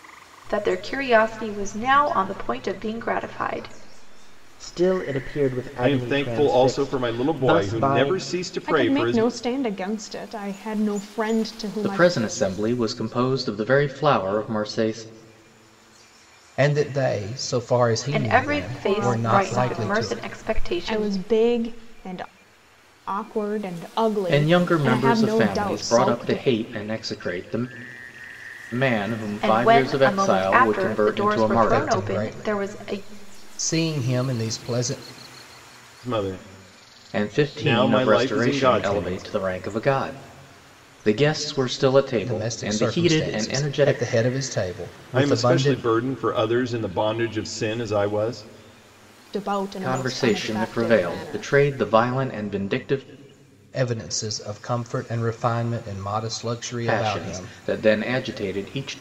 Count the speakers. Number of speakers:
6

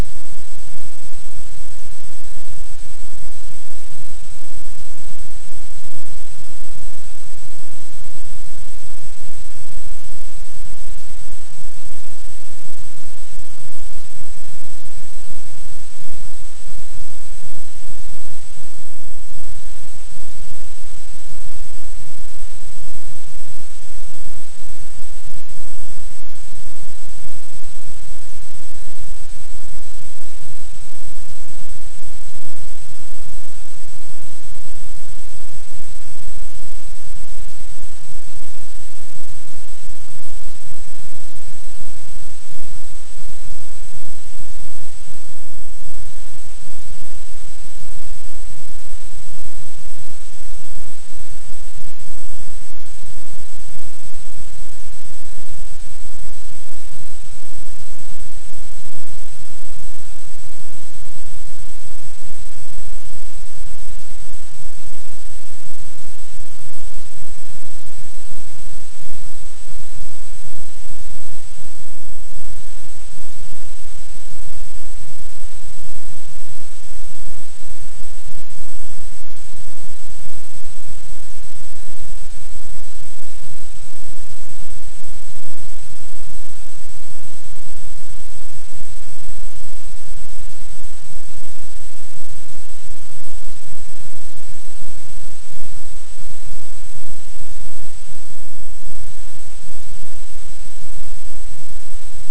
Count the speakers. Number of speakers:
0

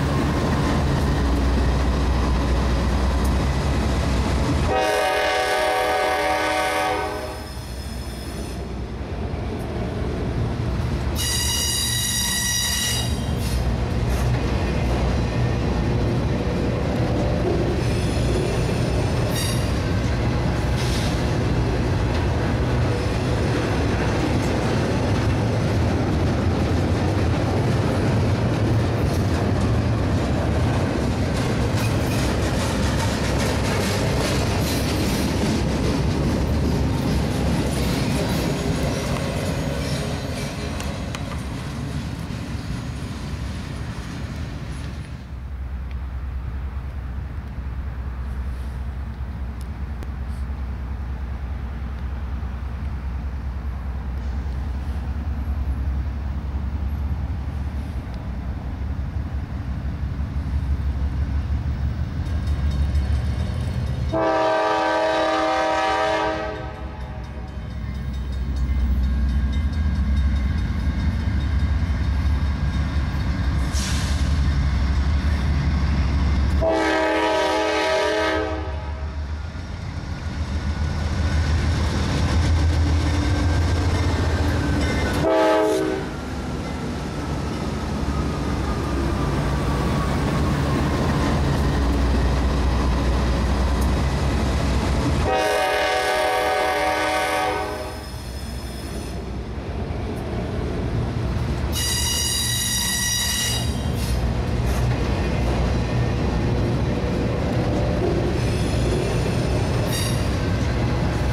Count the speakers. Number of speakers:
0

